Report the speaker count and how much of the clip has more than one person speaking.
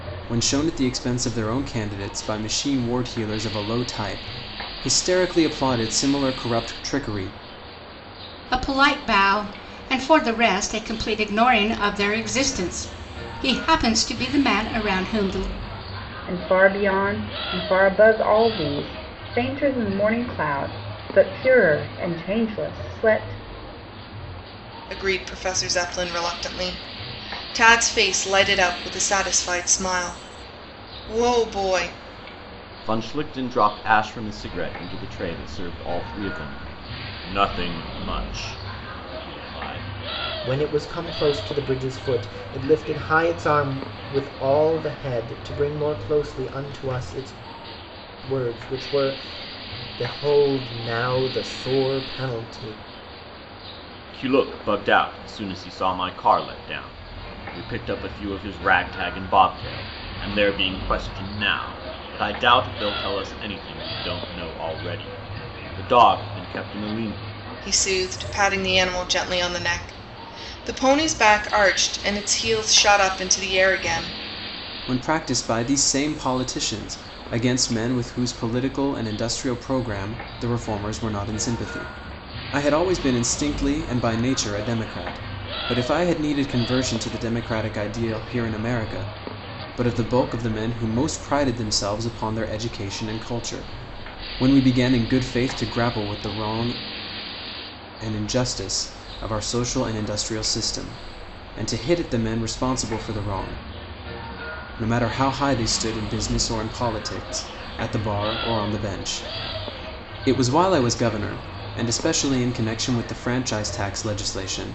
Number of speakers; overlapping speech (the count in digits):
6, no overlap